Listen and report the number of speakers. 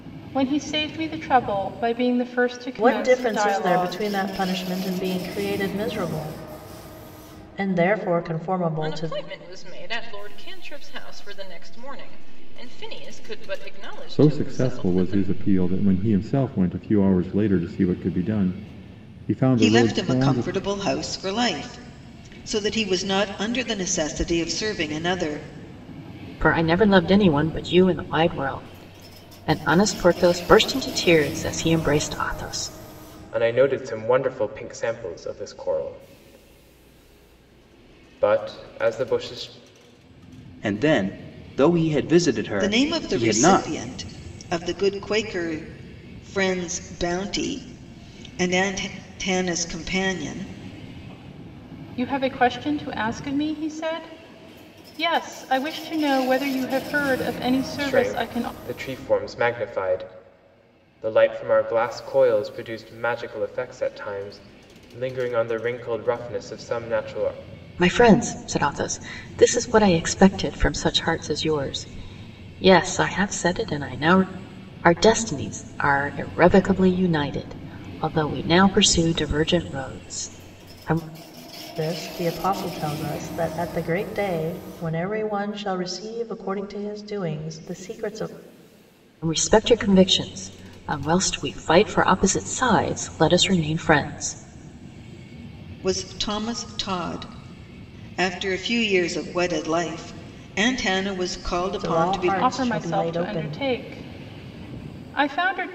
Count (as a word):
eight